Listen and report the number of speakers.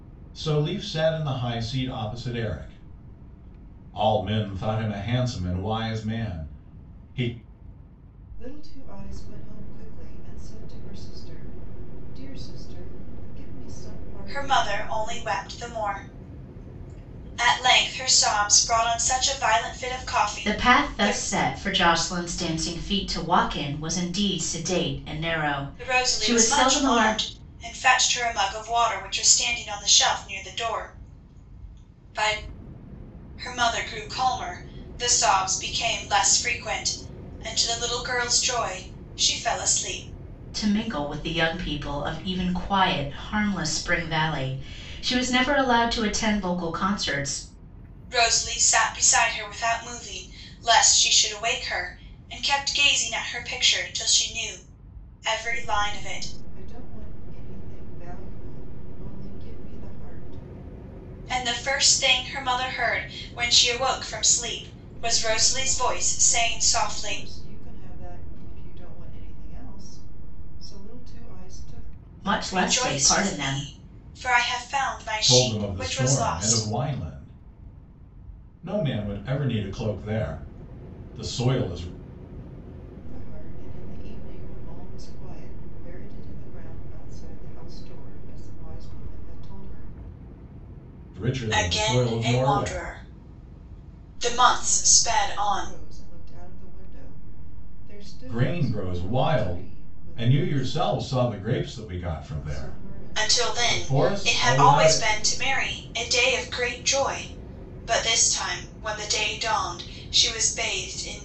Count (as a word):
four